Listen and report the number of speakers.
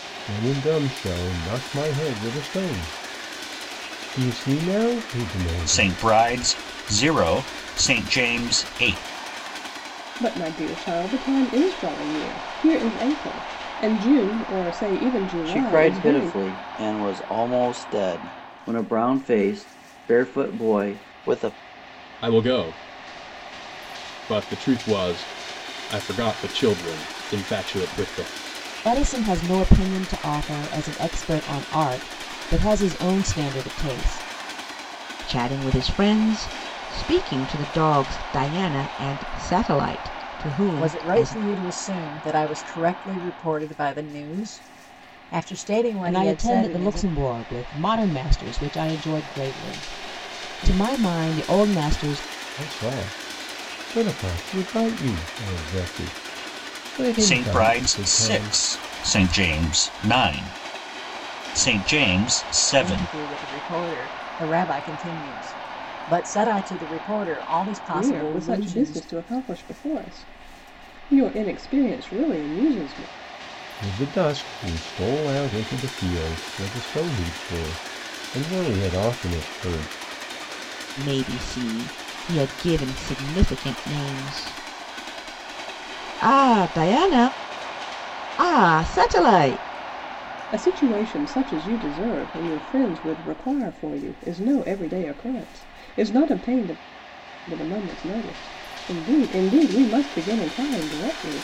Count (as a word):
eight